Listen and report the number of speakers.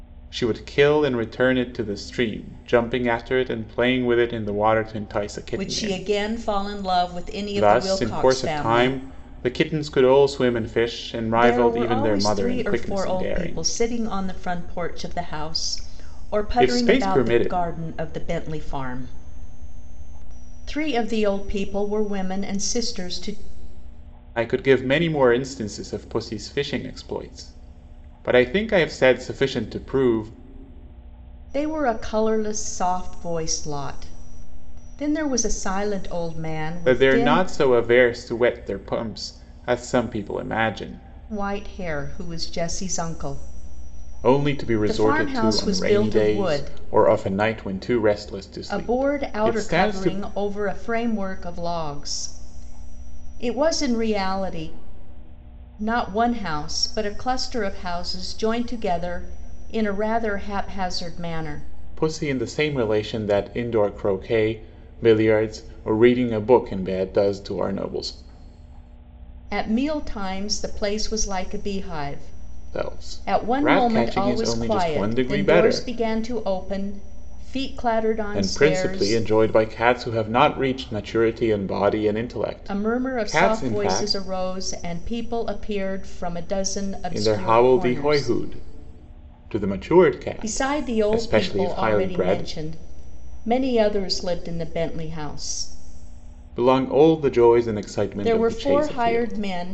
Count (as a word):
two